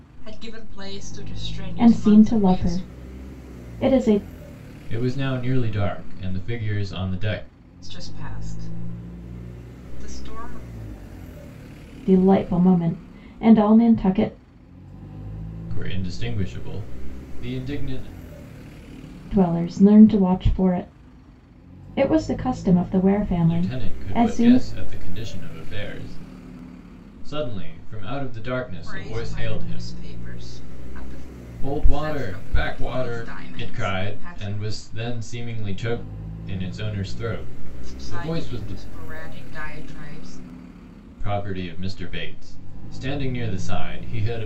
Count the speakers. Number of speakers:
3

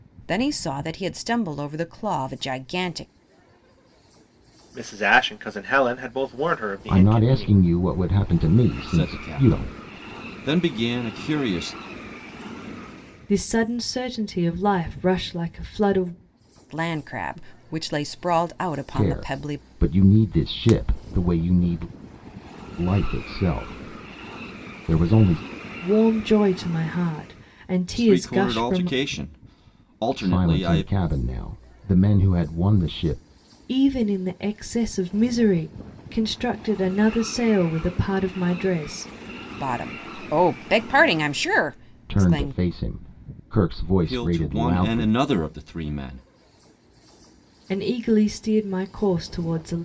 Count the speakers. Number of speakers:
5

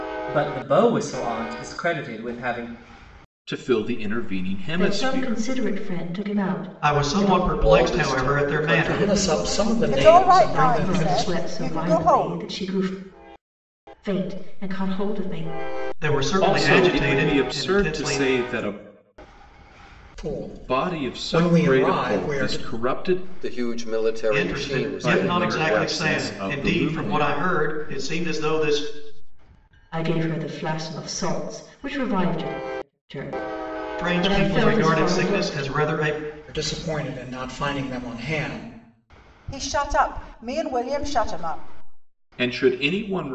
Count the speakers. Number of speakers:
9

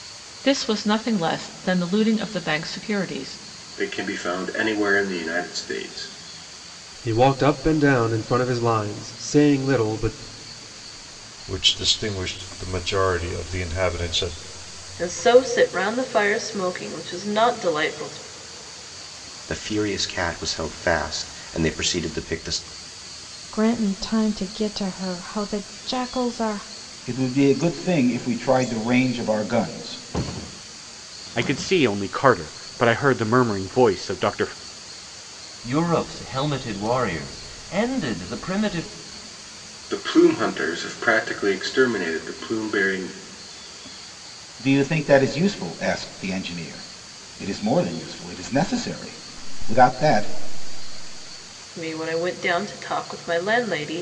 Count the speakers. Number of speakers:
10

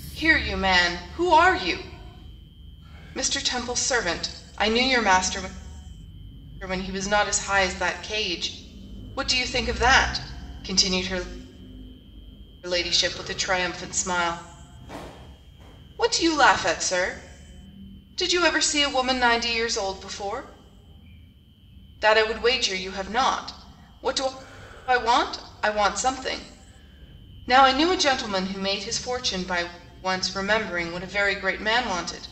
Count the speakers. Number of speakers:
1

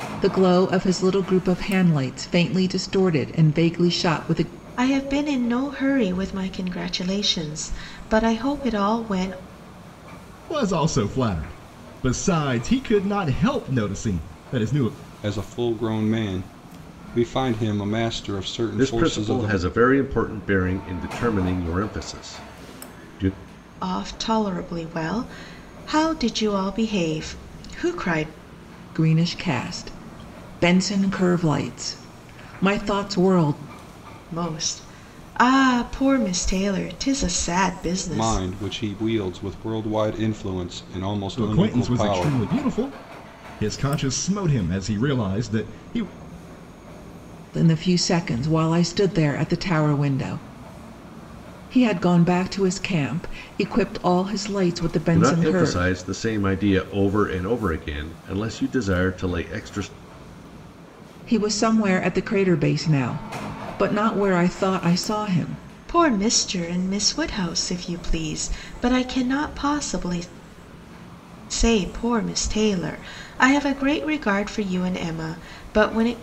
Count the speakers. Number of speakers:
5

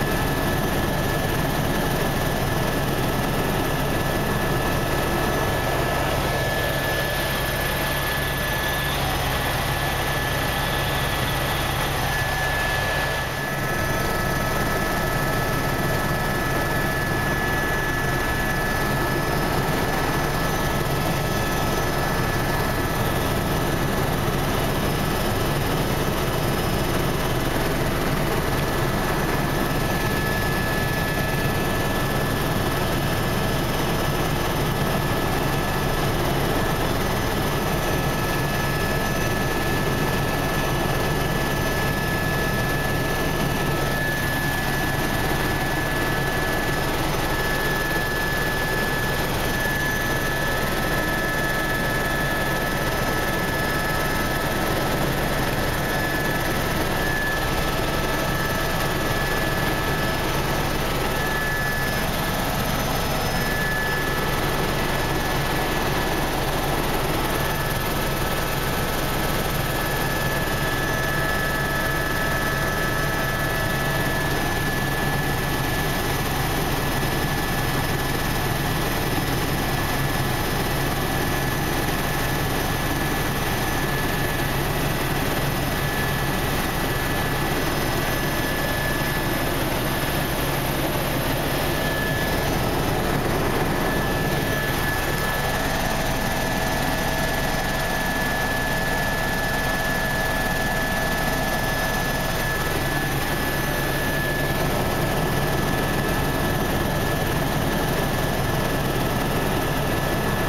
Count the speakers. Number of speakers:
0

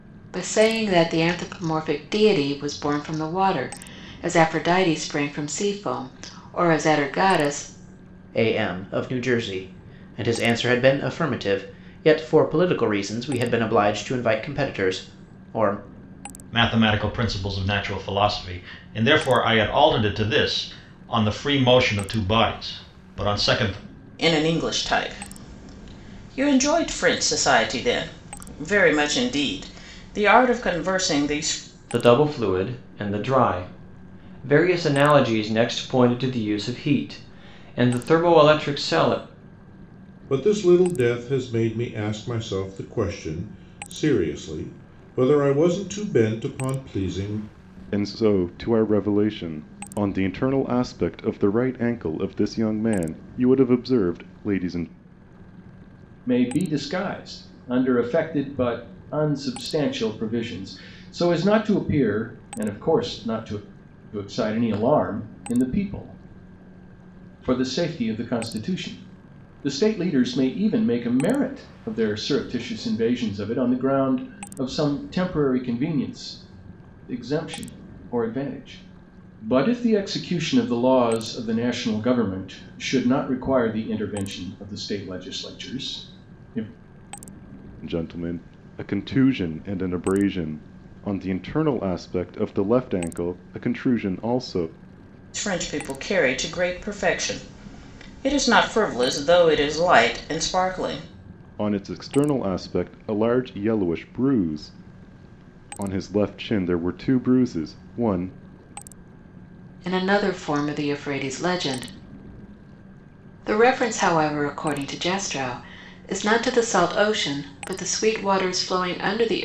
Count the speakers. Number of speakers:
8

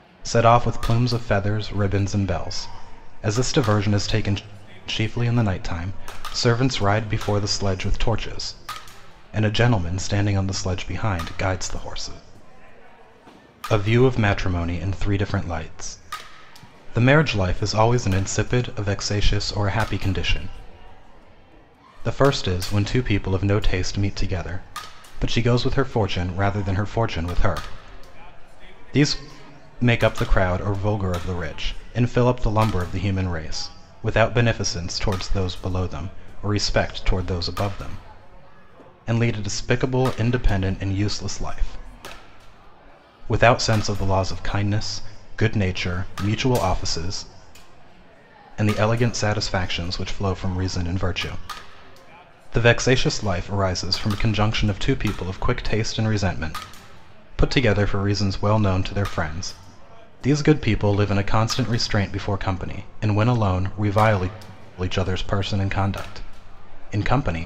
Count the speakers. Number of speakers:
1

